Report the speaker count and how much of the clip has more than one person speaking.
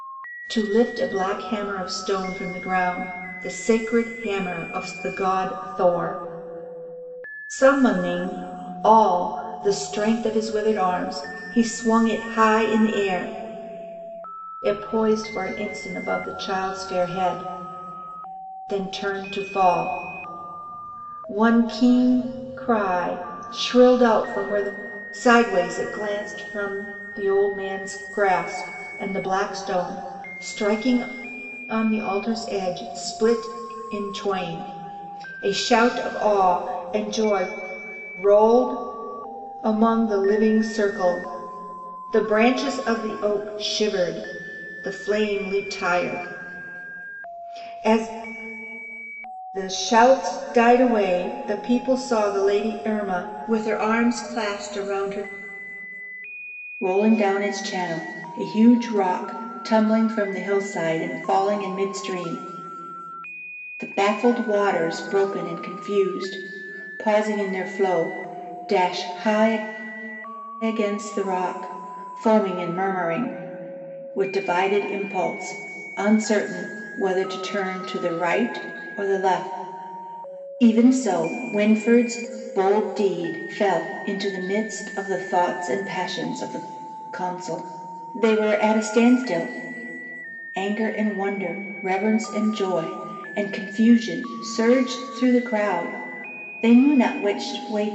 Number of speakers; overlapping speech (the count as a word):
one, no overlap